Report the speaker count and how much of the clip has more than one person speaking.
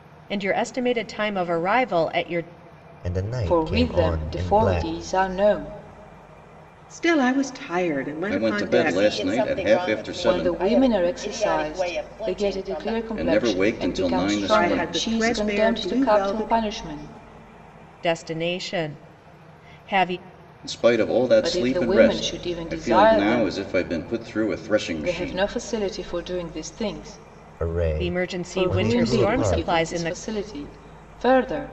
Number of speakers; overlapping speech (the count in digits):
6, about 46%